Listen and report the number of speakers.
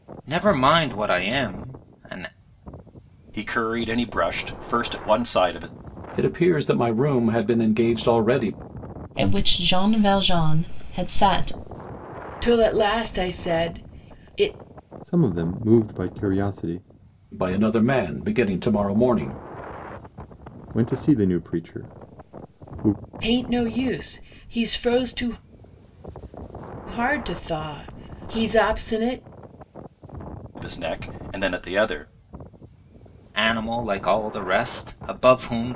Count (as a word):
six